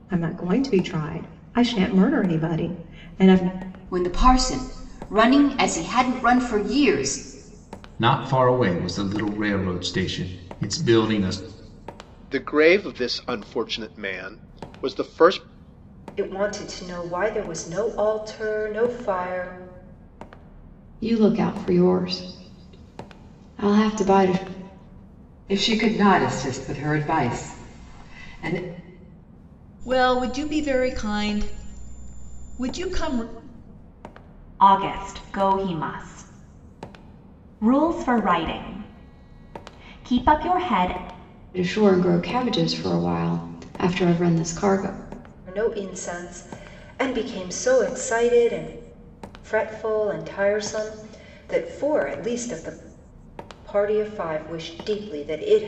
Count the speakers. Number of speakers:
nine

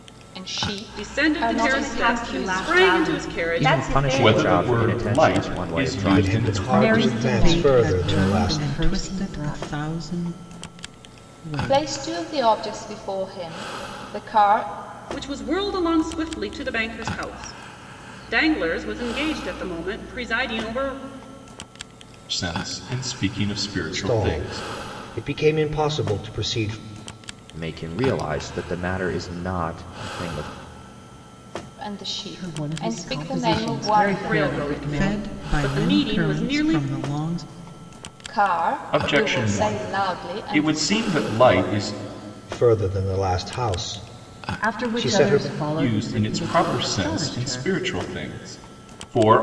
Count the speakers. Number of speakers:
eight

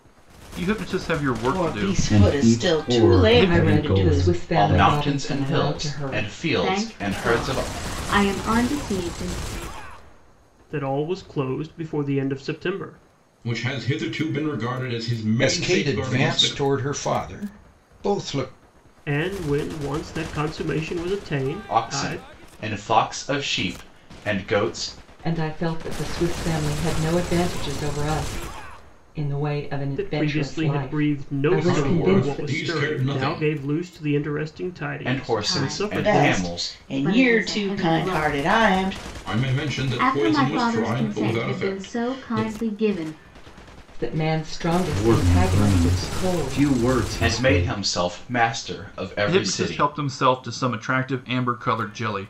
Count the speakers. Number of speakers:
nine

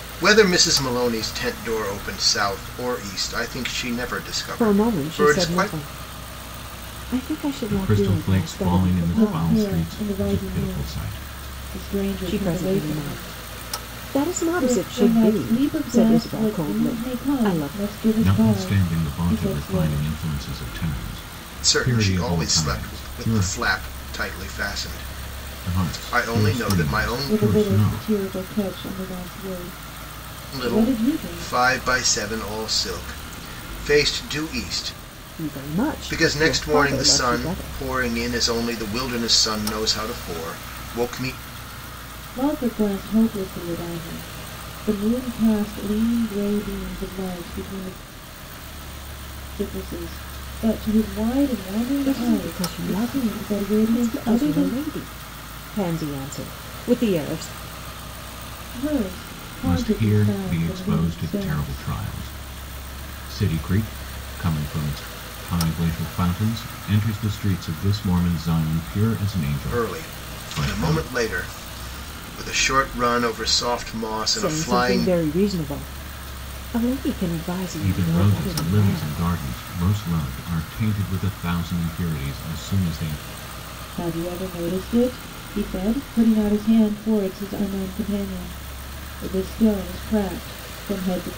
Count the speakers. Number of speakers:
four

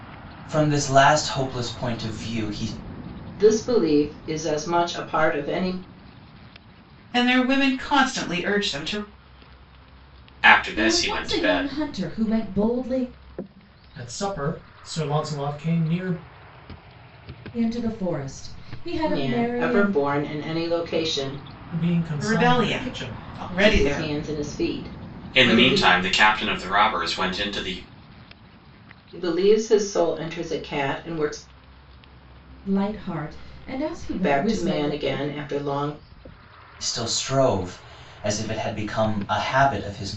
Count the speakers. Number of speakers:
six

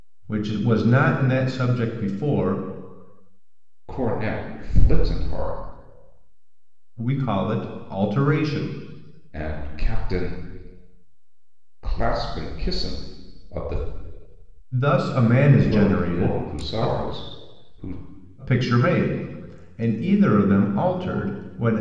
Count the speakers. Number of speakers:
two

